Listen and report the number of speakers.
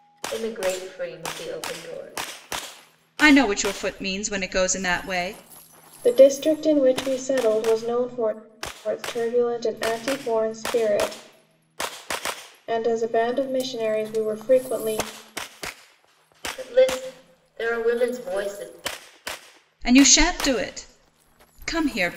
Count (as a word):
three